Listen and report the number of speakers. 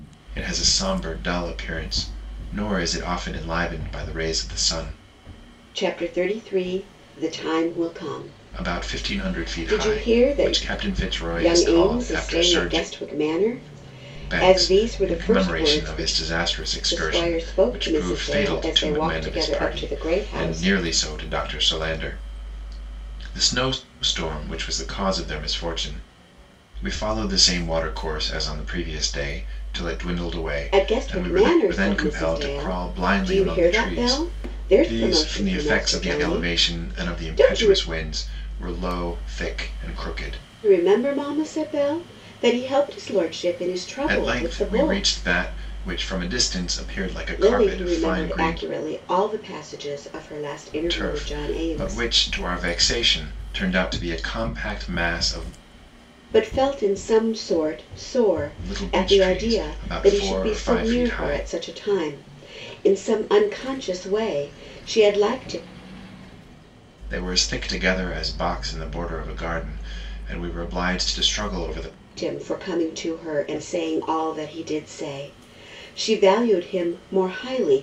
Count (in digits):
2